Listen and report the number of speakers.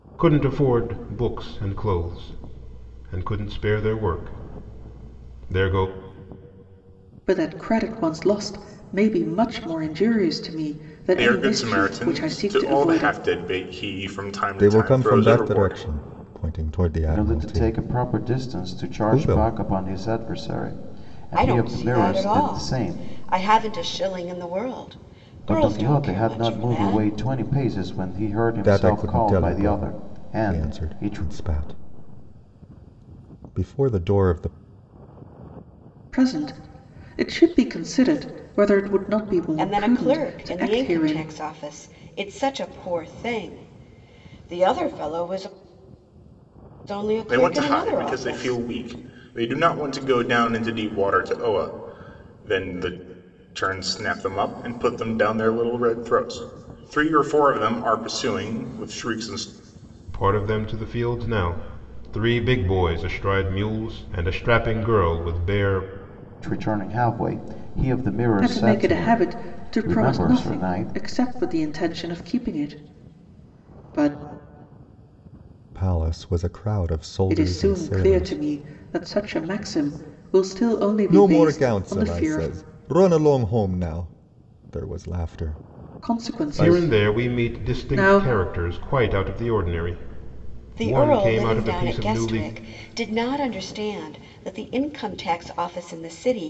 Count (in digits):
6